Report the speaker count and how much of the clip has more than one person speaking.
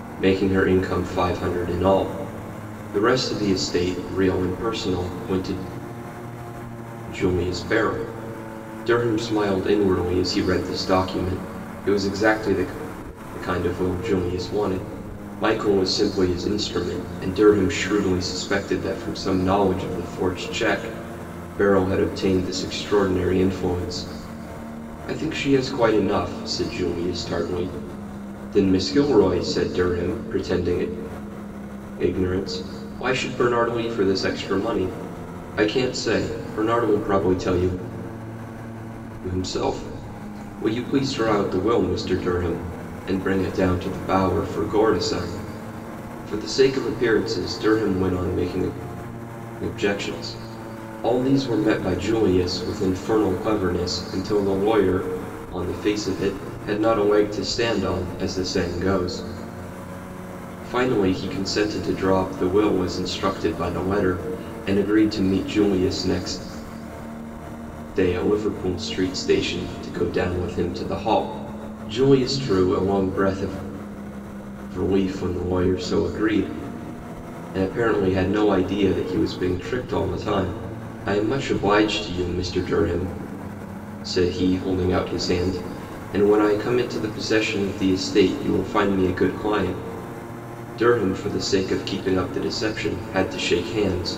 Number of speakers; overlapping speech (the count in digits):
1, no overlap